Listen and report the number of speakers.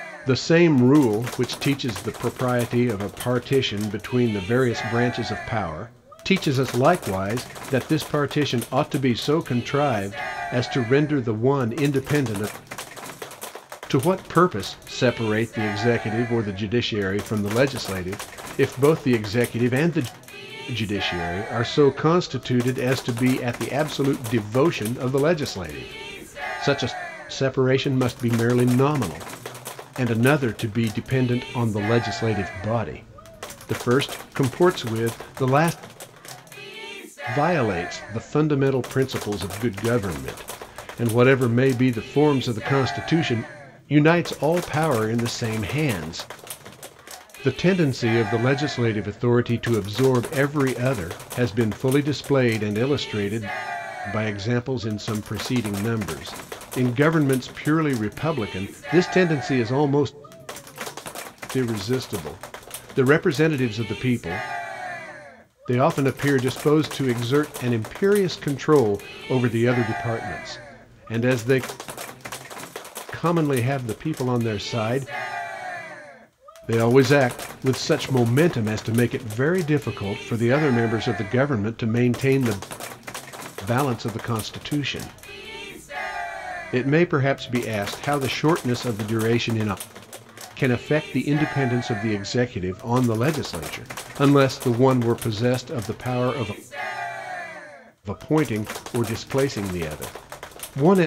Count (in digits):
1